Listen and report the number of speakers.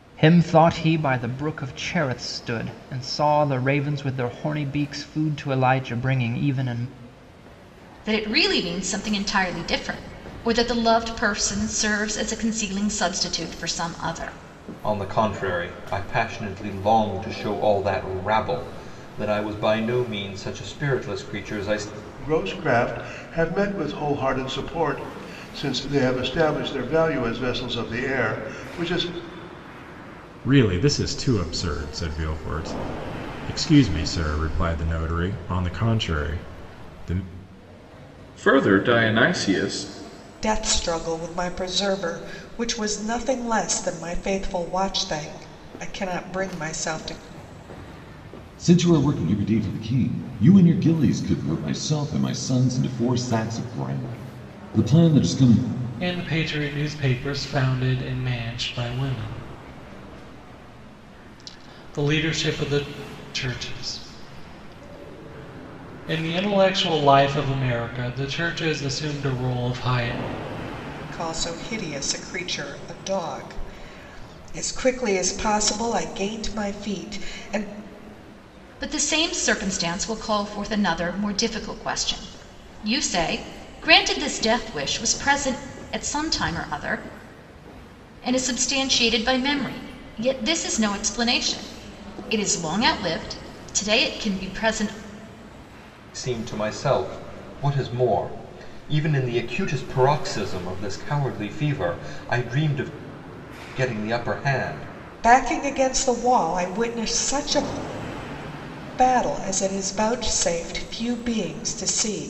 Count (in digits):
9